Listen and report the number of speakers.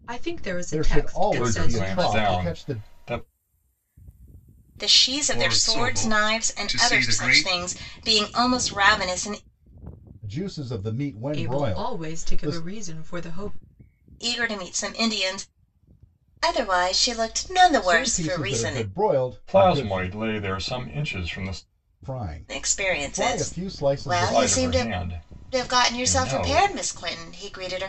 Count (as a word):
five